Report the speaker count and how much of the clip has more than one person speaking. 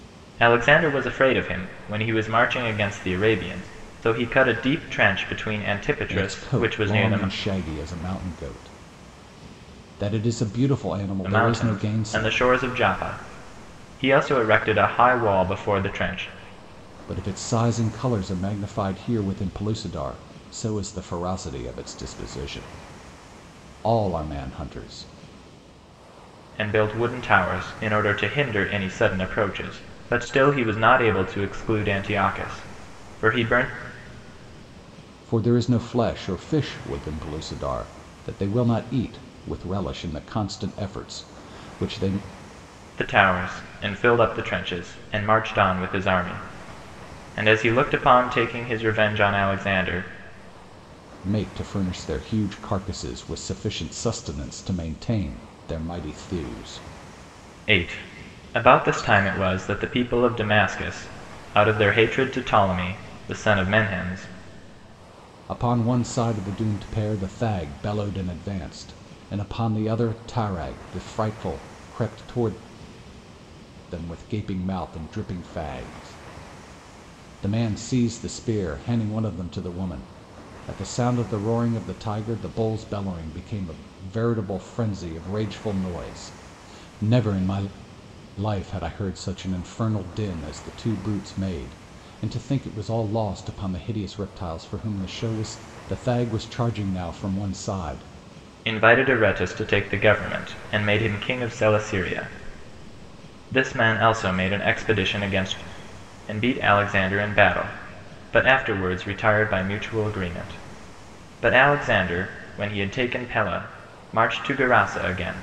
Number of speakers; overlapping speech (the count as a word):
two, about 2%